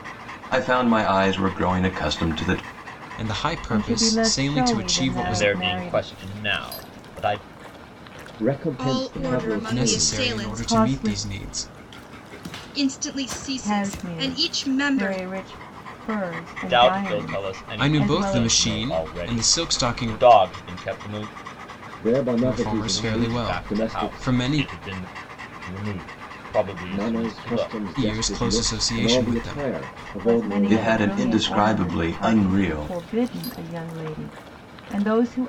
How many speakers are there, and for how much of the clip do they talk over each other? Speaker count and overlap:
6, about 50%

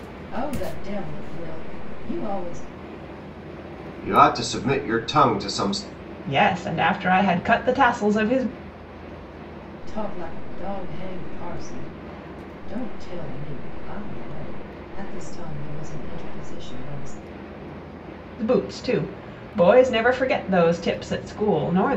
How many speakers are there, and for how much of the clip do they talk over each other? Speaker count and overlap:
3, no overlap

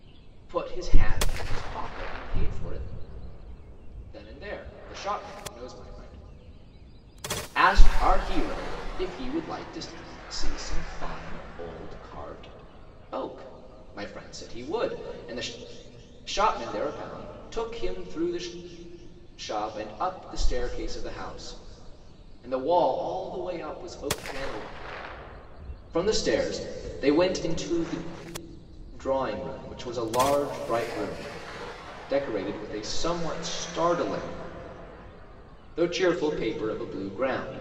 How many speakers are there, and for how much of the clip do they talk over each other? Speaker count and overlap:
1, no overlap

